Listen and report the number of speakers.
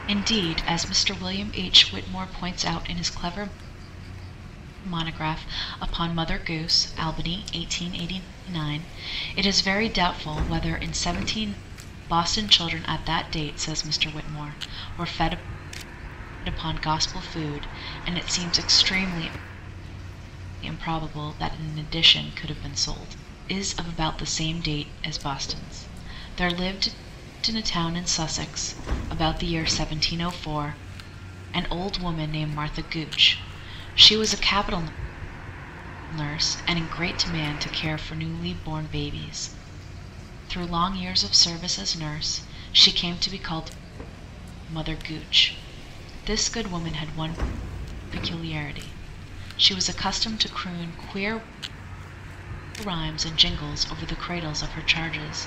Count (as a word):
one